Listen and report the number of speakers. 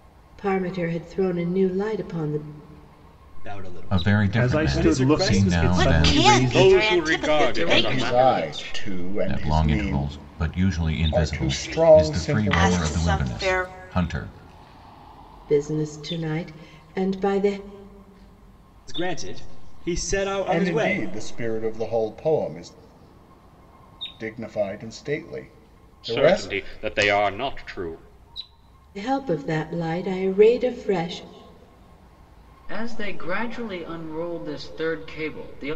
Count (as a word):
eight